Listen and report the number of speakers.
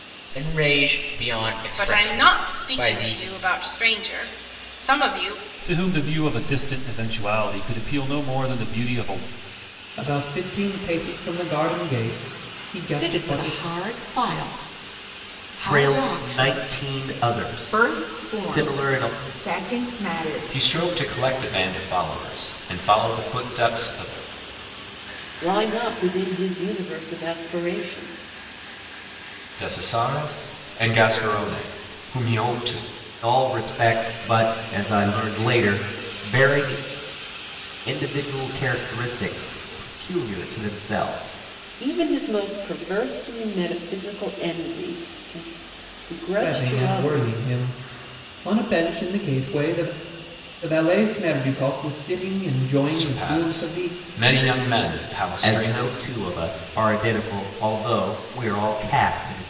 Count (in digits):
9